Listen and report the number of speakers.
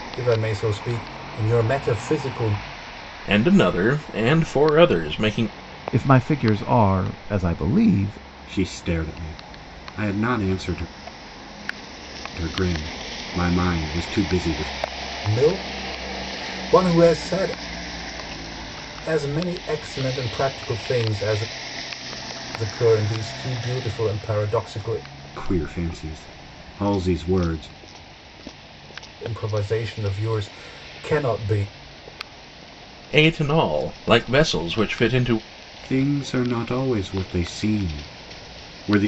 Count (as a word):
four